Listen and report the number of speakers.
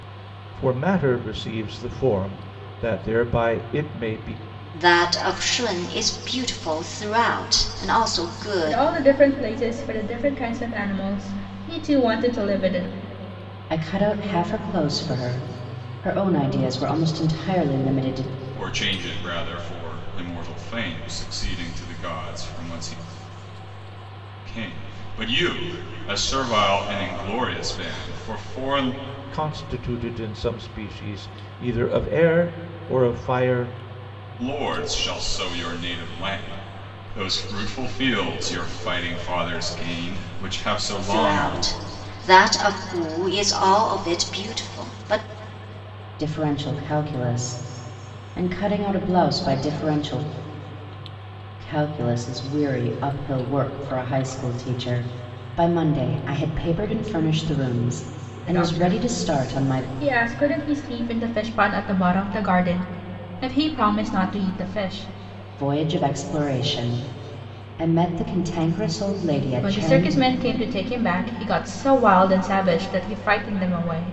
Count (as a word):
five